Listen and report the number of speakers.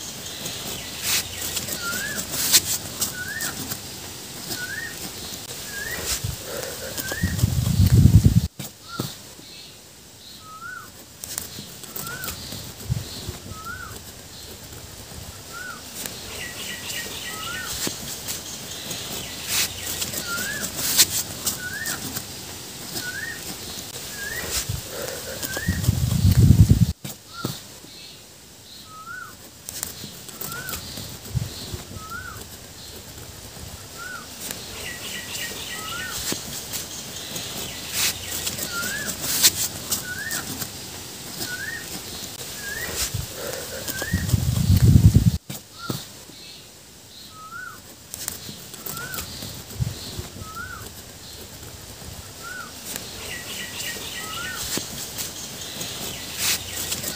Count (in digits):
0